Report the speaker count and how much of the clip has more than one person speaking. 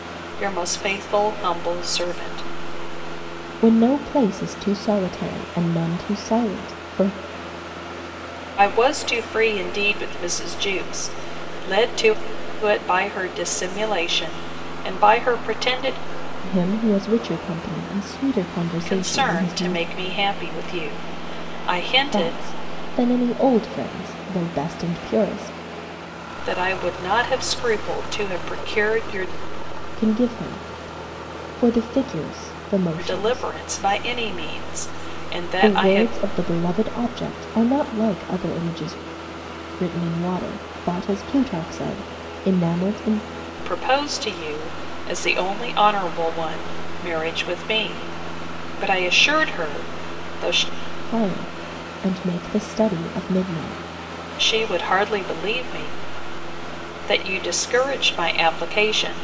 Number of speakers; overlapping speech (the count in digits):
2, about 4%